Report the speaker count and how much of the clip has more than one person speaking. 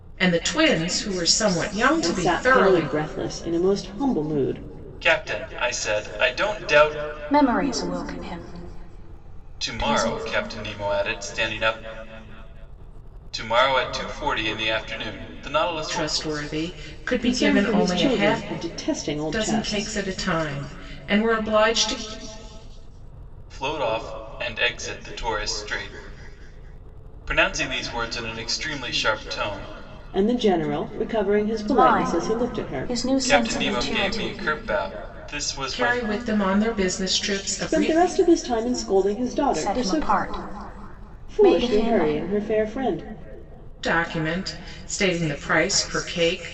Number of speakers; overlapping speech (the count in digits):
4, about 18%